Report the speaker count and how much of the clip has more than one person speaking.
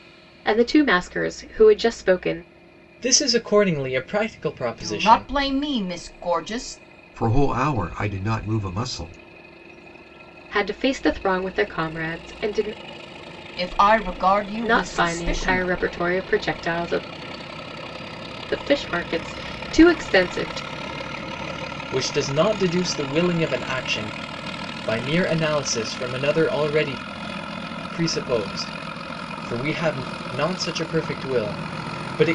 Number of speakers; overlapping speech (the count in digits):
4, about 5%